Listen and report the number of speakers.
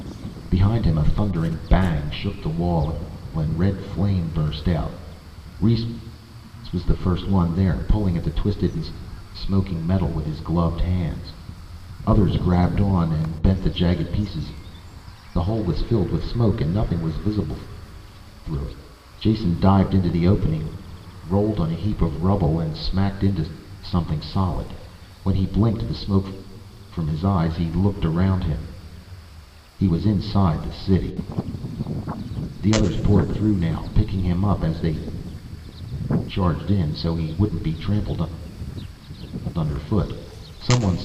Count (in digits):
1